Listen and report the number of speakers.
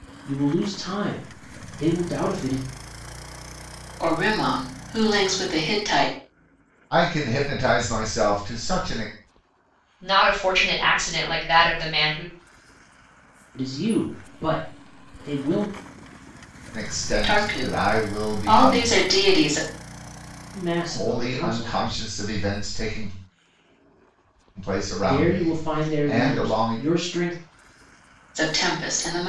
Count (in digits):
4